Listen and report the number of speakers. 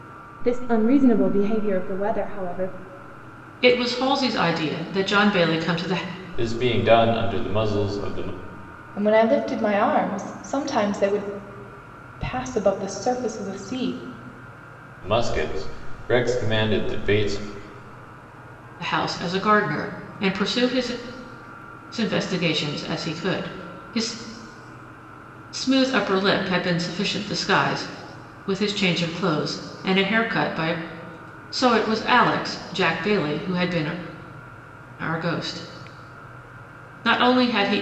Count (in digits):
4